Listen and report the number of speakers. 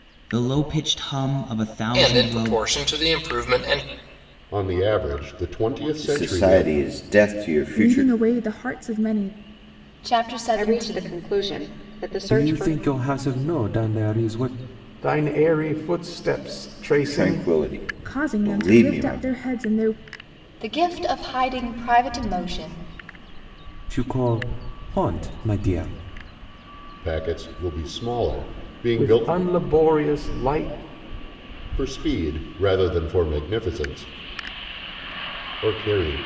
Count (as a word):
nine